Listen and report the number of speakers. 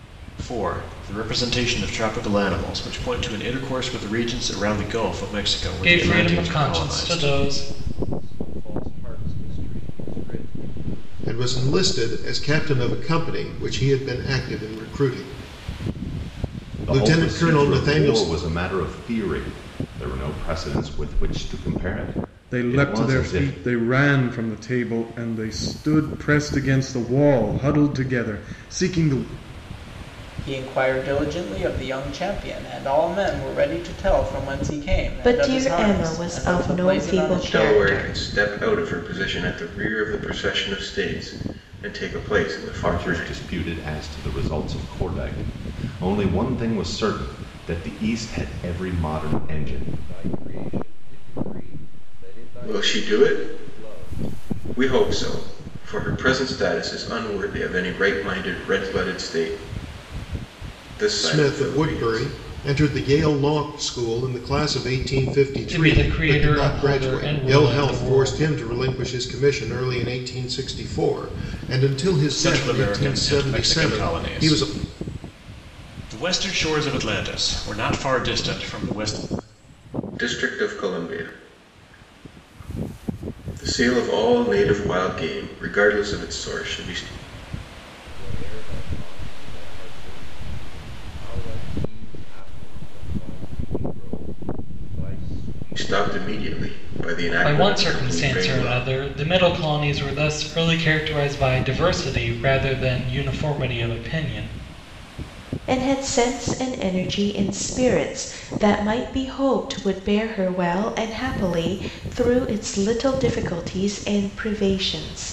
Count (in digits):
9